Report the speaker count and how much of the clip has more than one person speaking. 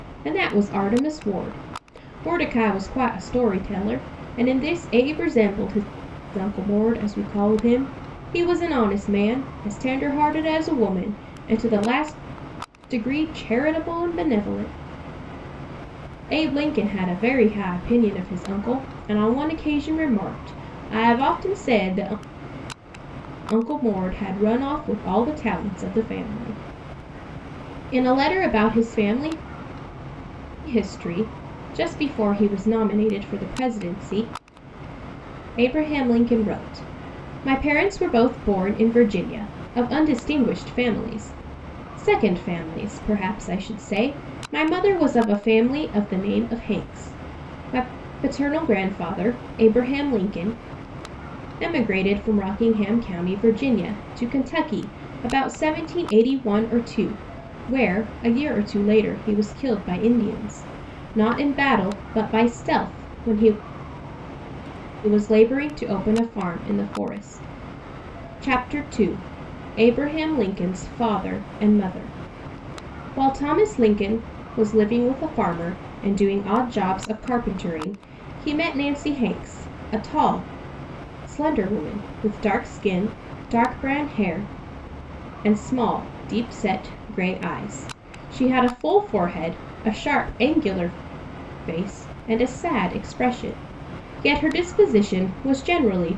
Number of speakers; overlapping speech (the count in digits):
1, no overlap